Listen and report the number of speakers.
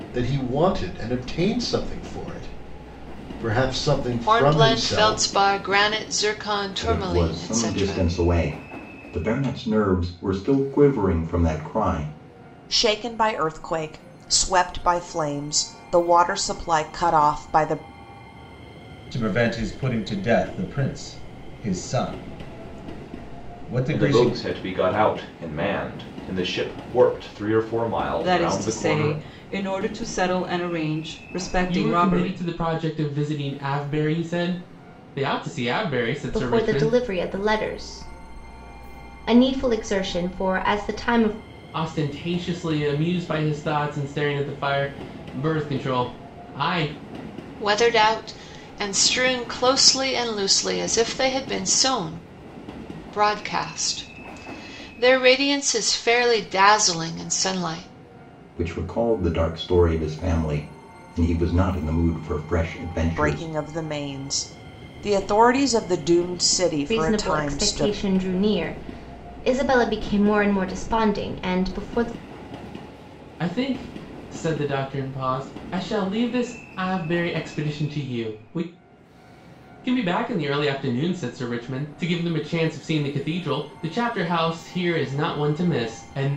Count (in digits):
9